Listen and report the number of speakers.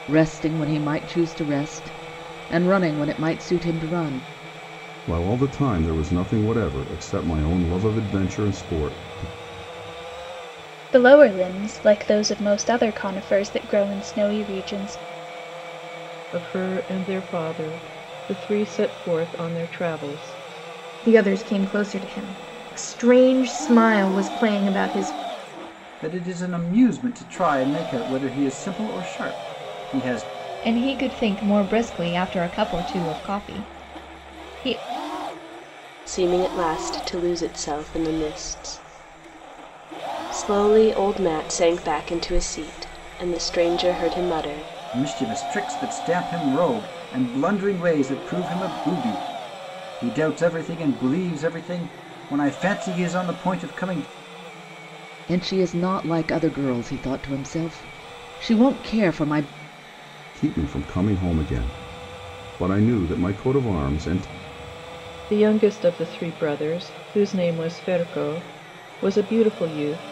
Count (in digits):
8